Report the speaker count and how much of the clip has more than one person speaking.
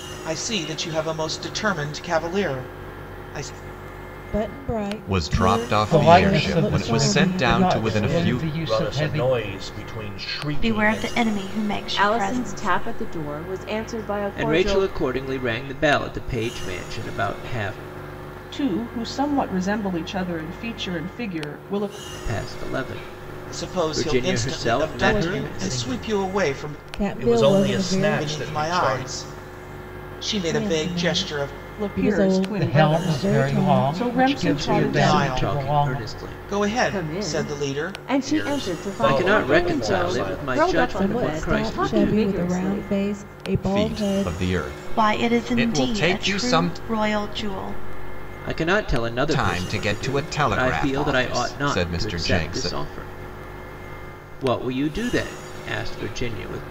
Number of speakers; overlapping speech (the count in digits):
9, about 52%